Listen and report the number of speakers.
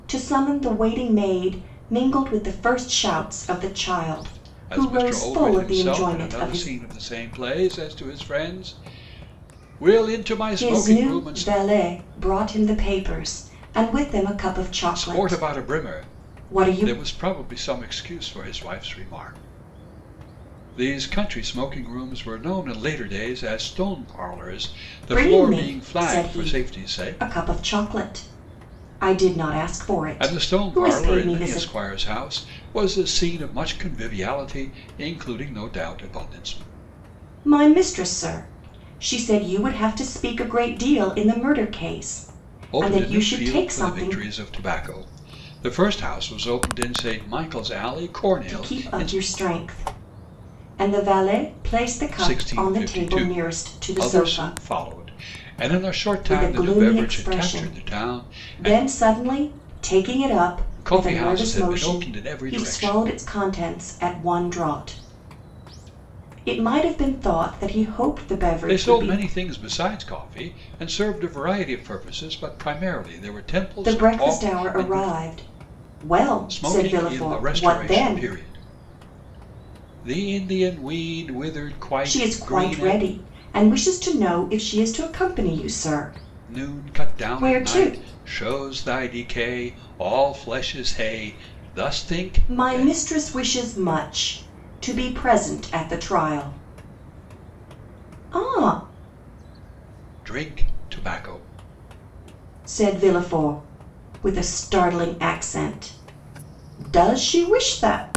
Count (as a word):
two